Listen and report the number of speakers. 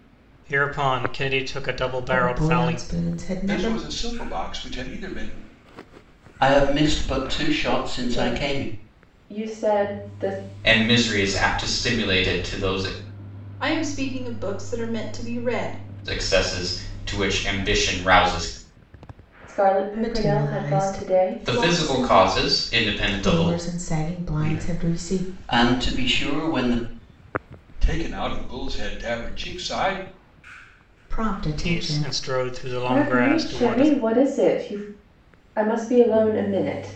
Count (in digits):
7